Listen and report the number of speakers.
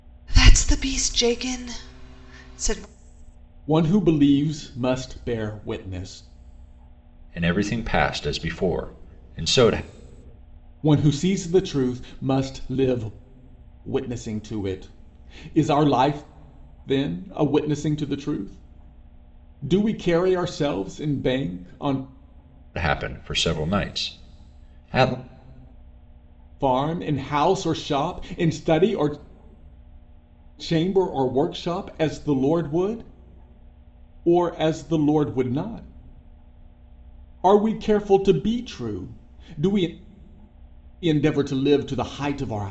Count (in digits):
3